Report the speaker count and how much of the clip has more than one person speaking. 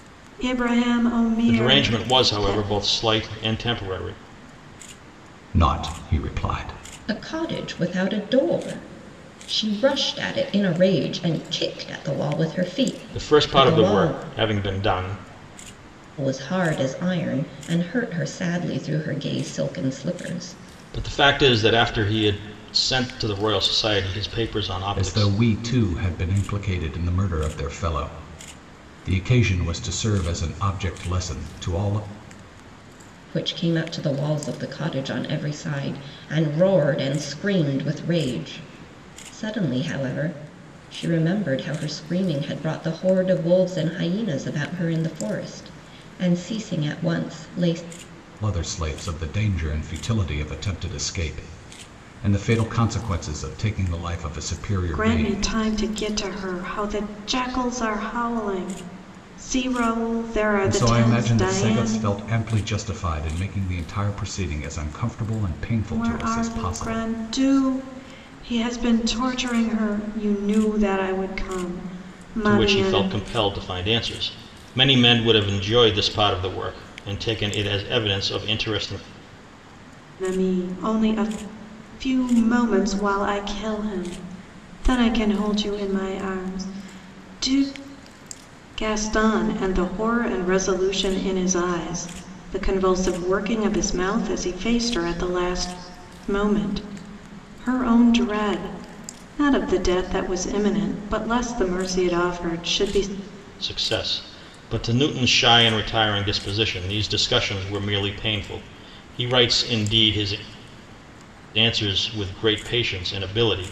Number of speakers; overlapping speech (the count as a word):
four, about 6%